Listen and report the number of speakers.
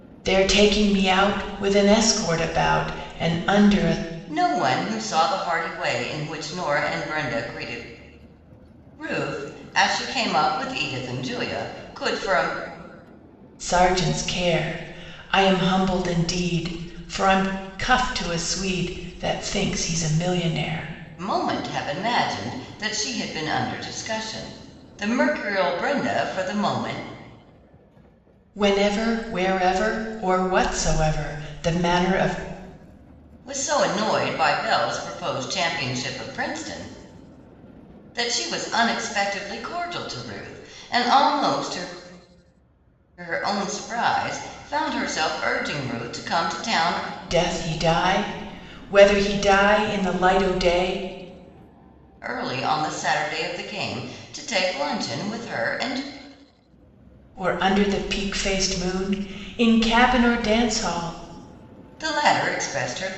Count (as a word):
two